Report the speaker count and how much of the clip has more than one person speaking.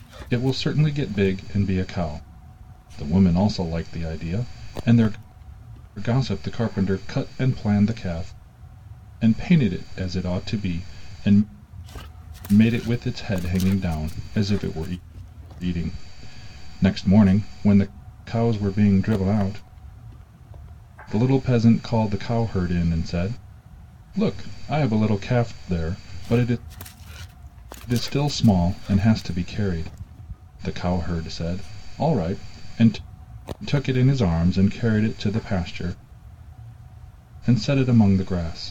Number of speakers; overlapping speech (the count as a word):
one, no overlap